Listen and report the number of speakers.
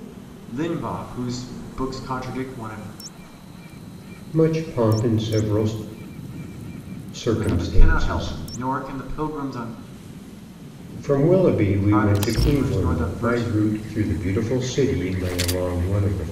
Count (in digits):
2